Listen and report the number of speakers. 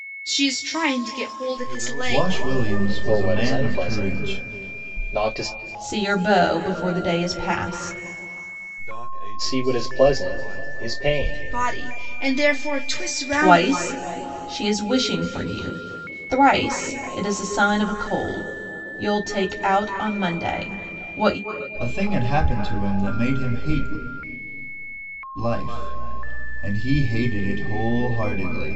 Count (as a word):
five